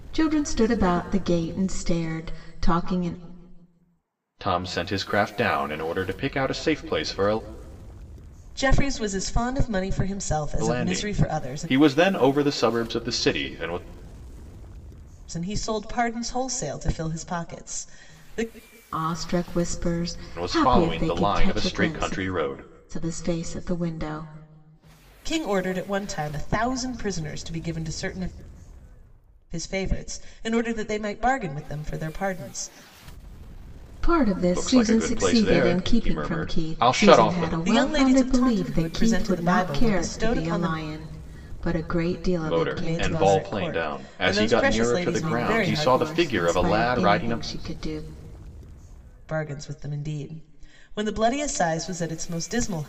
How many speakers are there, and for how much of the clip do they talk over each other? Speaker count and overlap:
3, about 27%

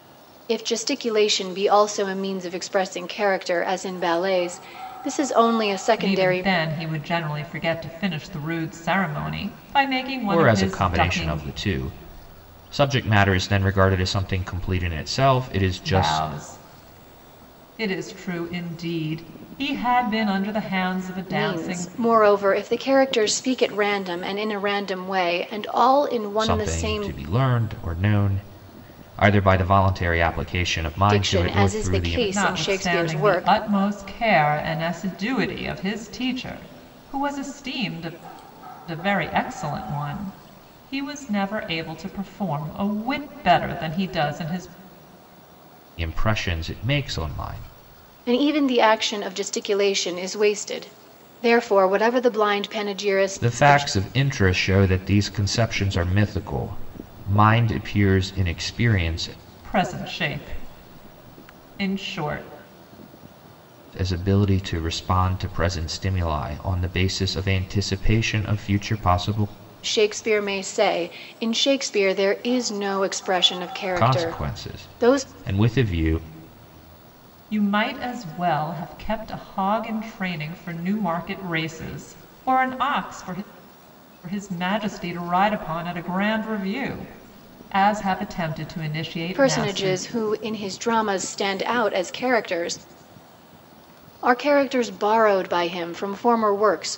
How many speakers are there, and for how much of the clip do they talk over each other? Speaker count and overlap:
3, about 9%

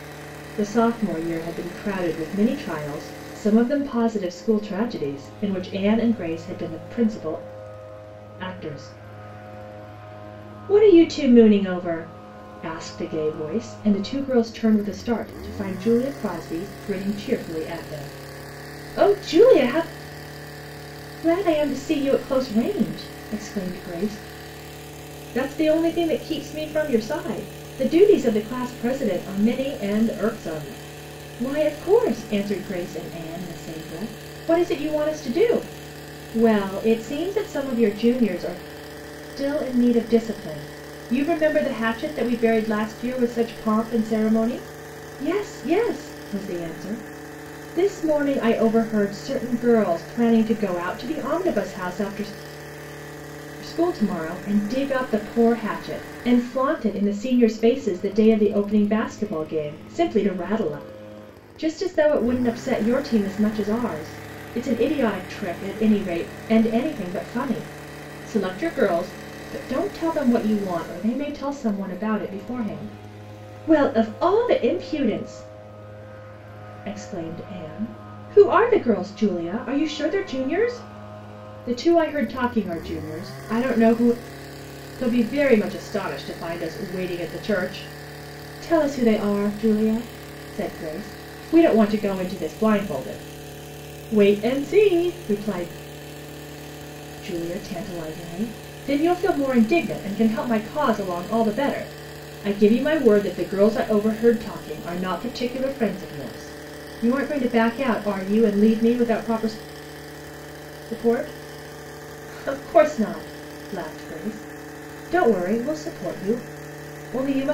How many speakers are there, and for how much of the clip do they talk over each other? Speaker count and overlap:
1, no overlap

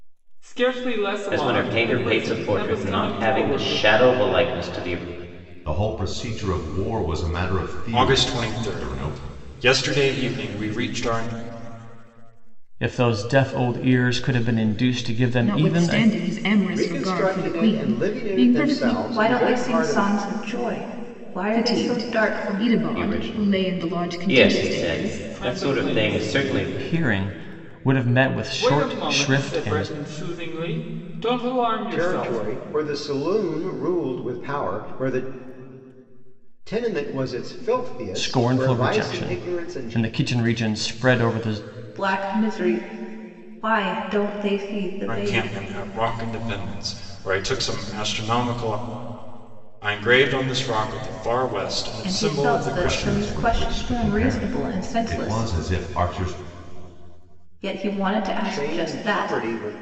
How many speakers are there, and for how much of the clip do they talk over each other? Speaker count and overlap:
8, about 39%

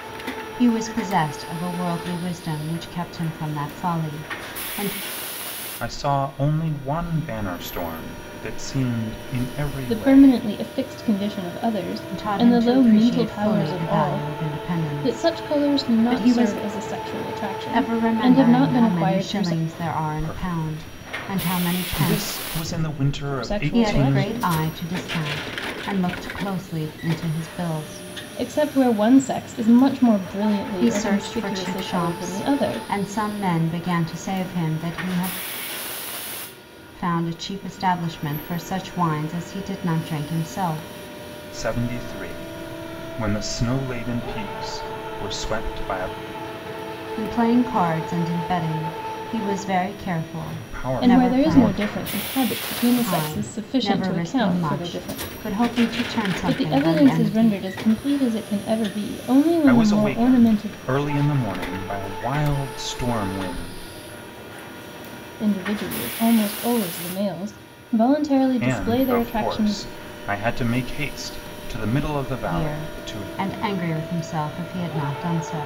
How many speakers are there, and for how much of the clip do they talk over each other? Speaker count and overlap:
3, about 26%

